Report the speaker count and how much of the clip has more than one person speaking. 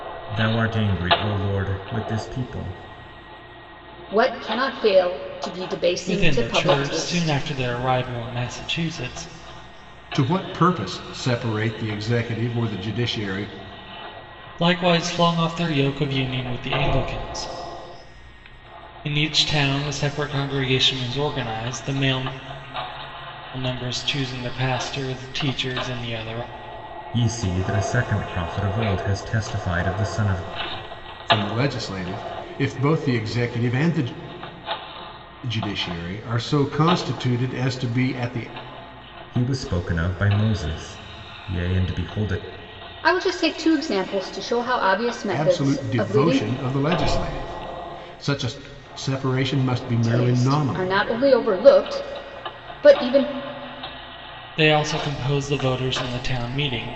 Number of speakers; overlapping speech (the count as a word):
four, about 6%